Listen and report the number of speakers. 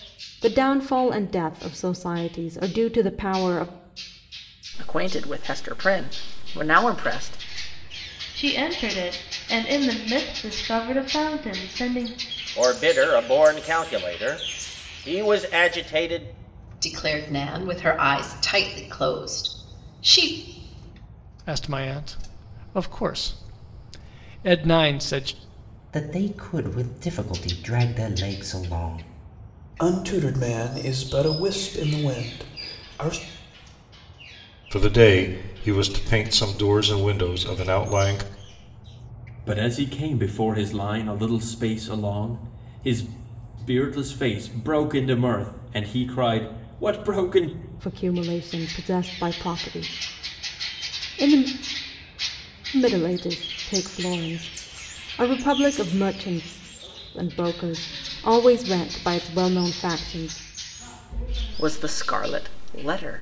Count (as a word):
ten